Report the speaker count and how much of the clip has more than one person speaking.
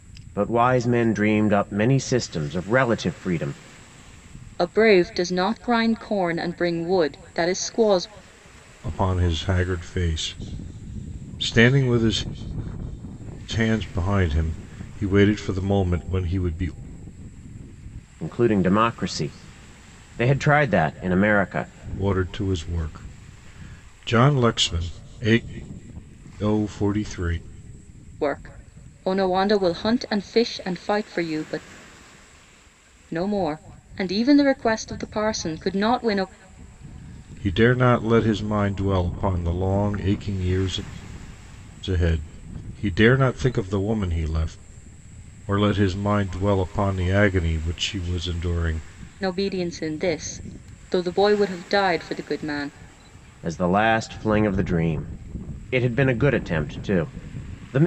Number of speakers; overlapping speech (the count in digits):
3, no overlap